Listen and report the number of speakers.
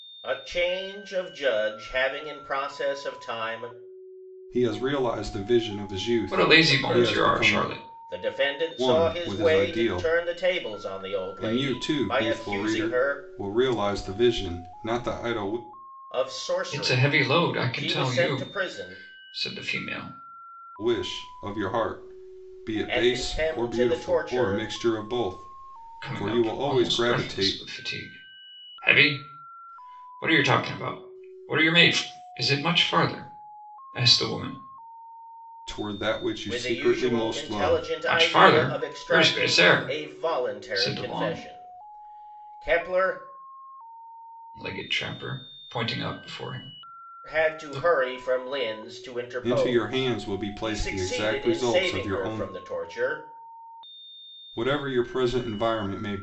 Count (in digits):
3